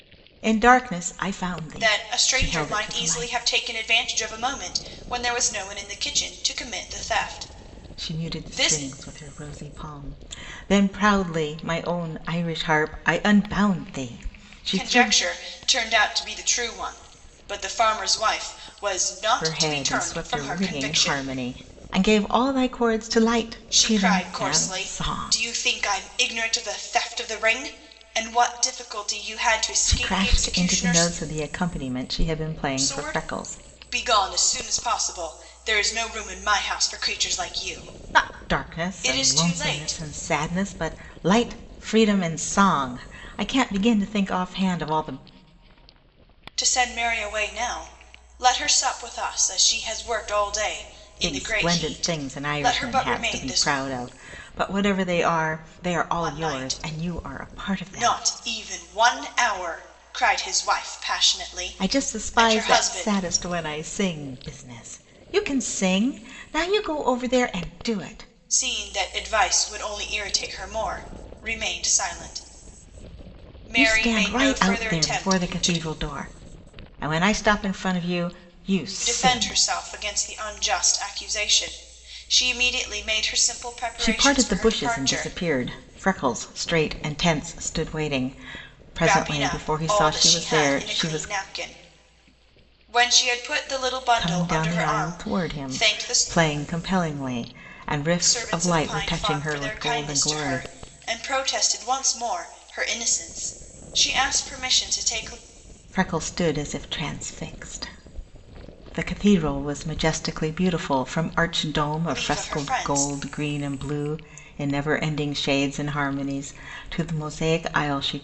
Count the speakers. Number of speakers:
2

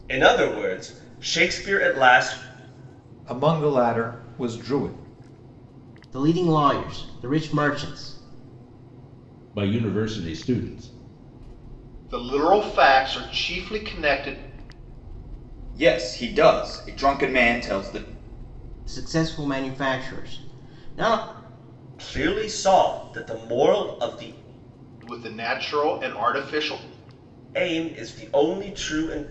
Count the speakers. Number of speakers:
6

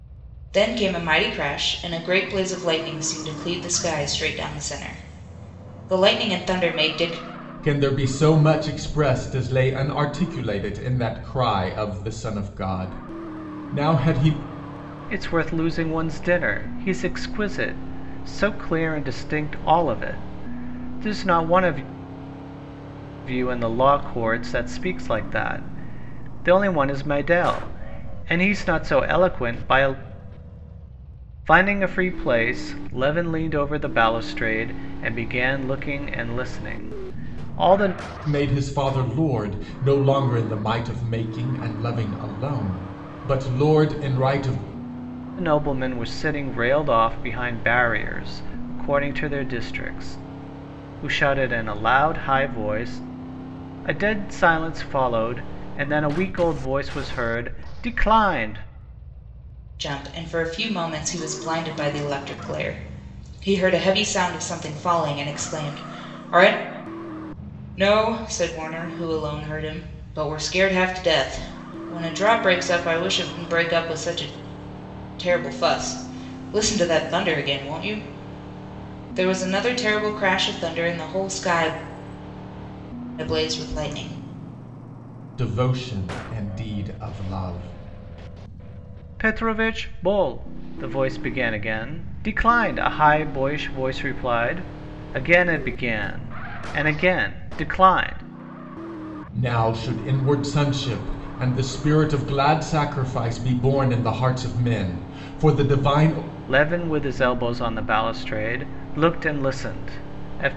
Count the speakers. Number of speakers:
3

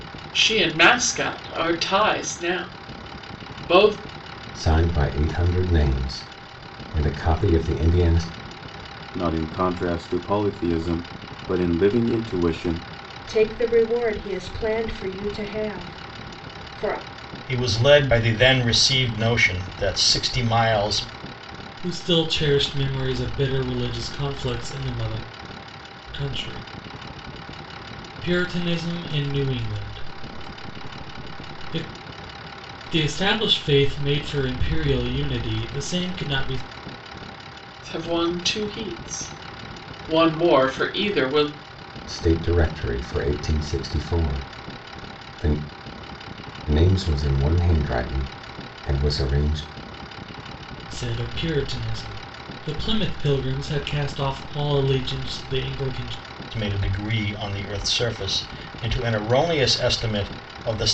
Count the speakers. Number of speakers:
6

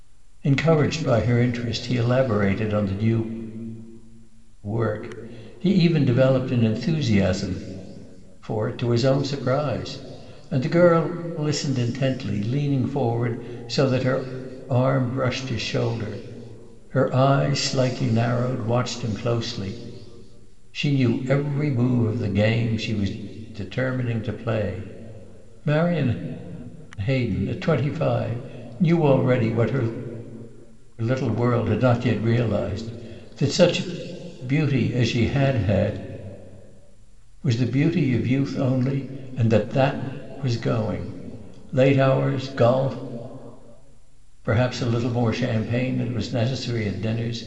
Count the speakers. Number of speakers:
1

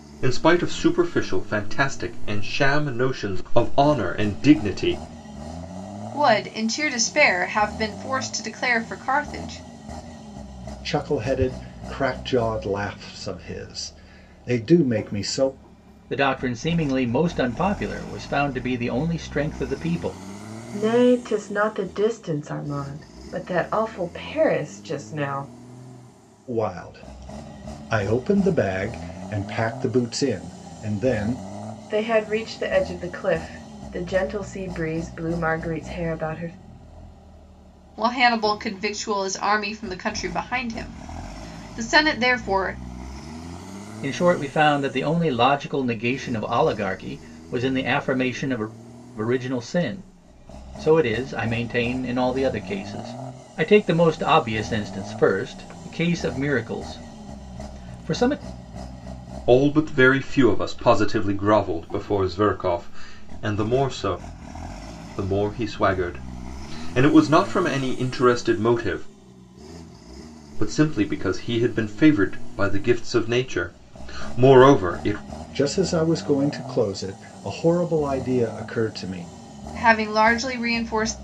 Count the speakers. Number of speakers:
5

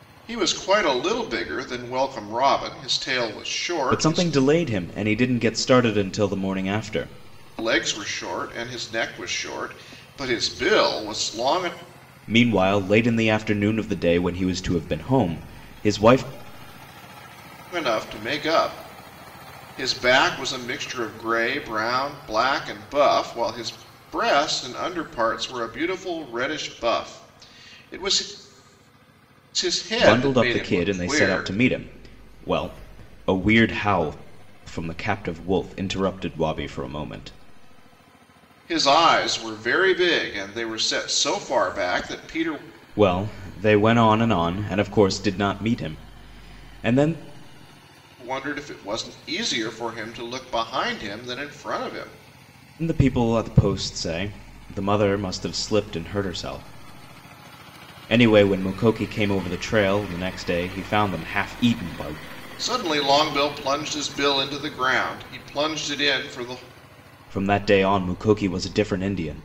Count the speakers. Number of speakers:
2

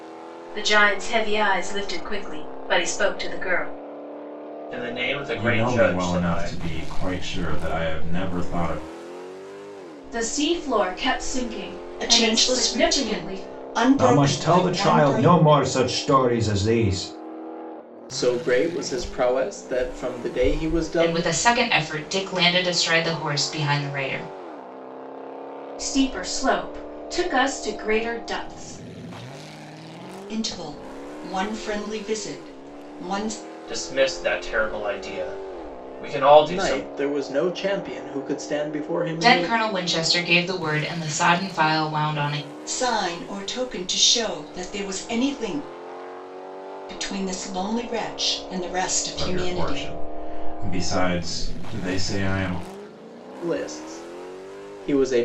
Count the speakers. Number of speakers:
8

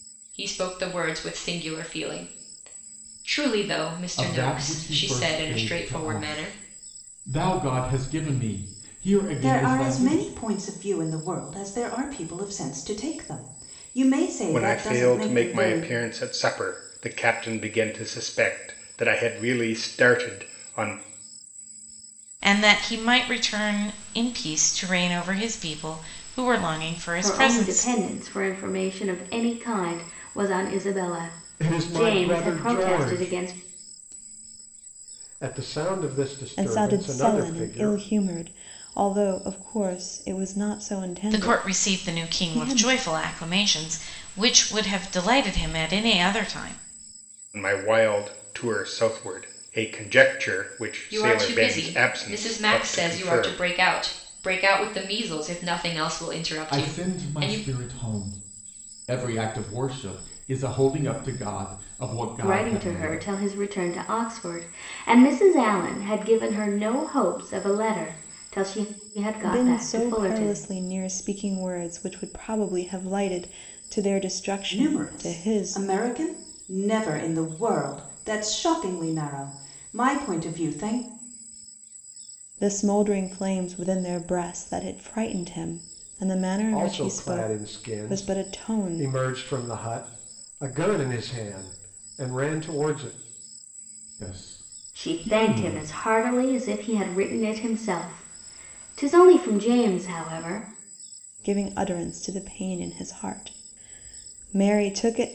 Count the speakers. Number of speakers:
8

